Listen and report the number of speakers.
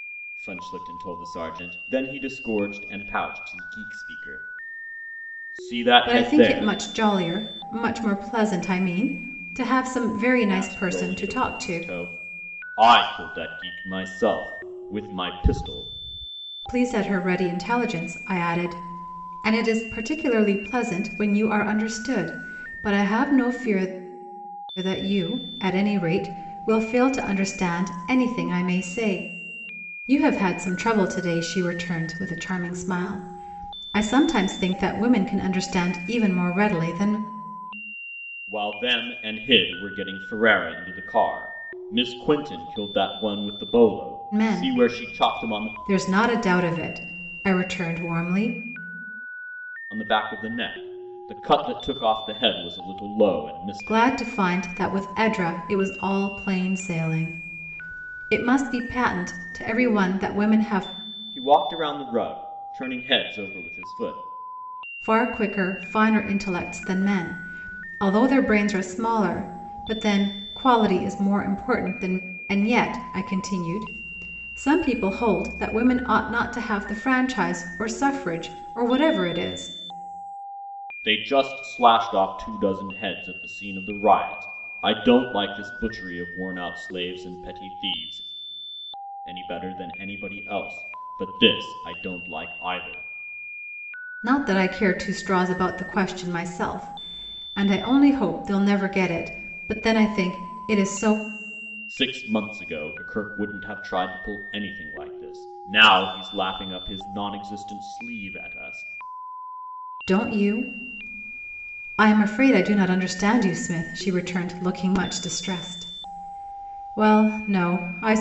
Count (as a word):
two